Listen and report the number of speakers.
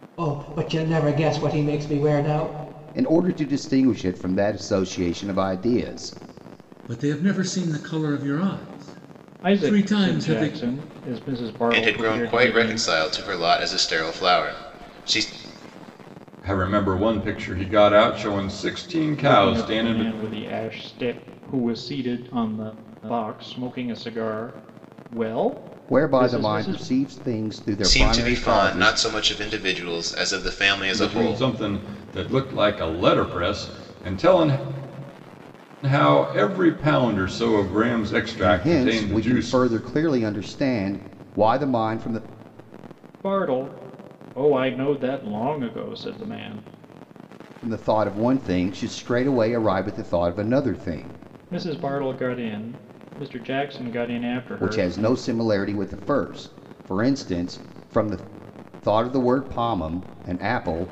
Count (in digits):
6